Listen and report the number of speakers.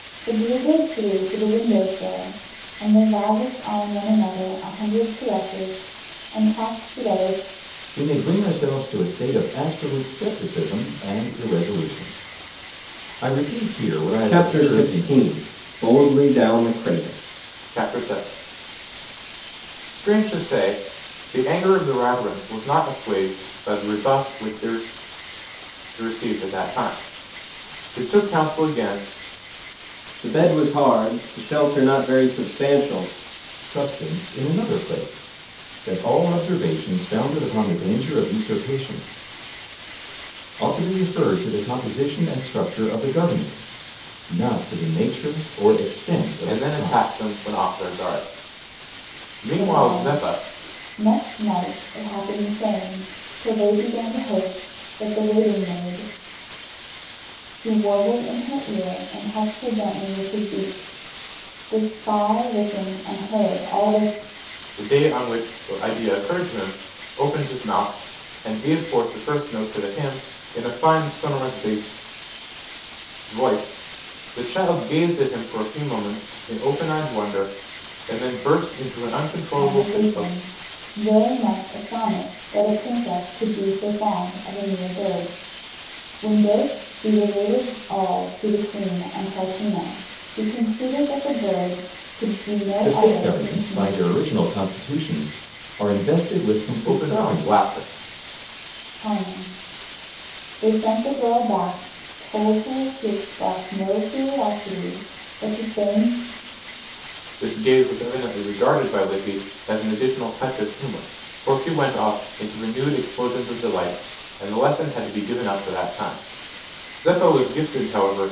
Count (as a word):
four